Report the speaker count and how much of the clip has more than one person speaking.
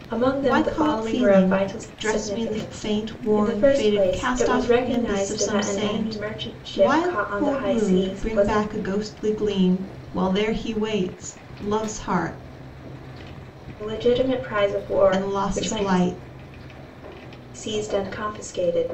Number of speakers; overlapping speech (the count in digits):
2, about 46%